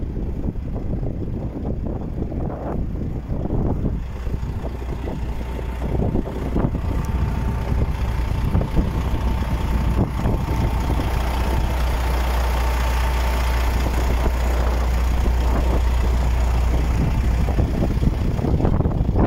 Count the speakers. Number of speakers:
zero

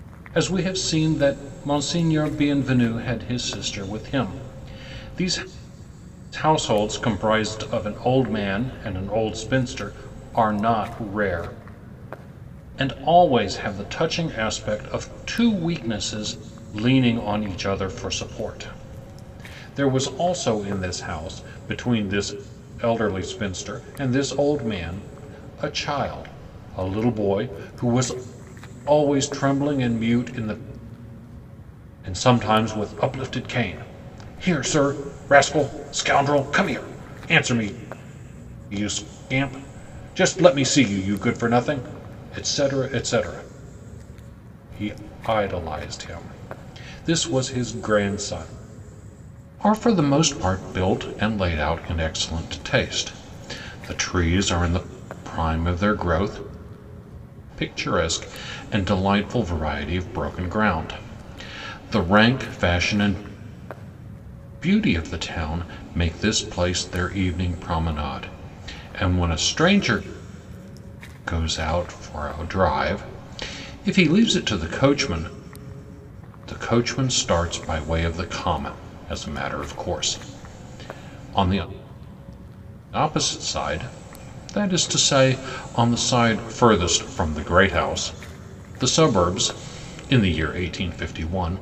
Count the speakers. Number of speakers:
one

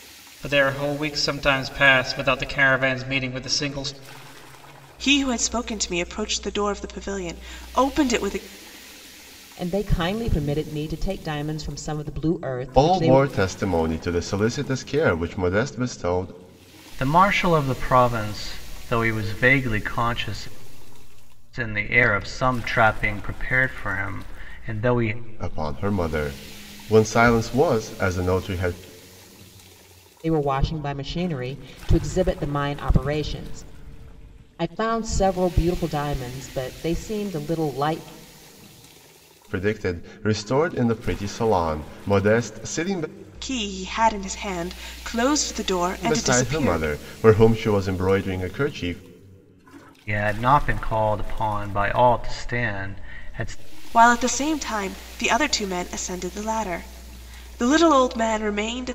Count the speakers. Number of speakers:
five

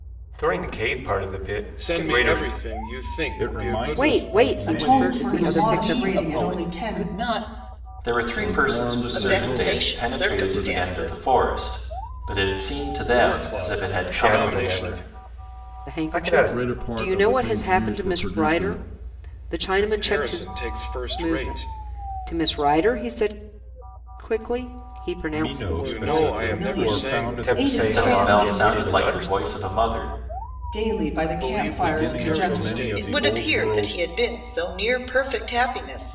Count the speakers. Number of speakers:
nine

